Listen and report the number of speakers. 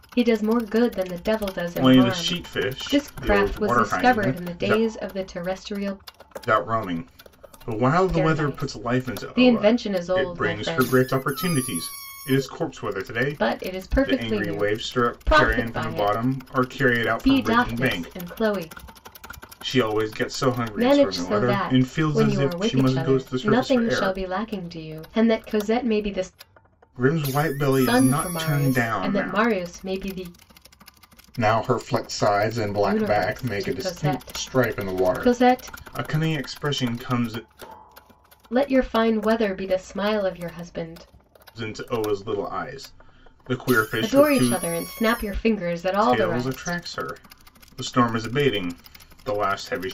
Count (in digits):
2